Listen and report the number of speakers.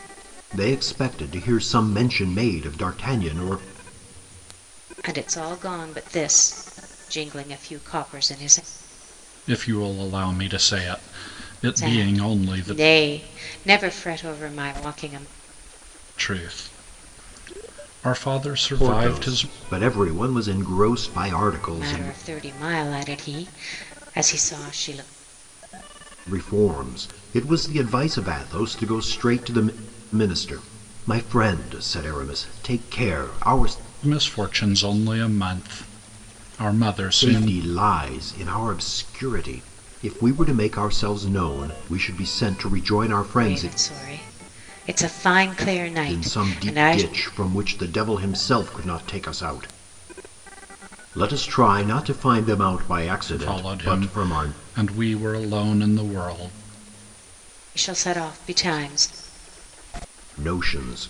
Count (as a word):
three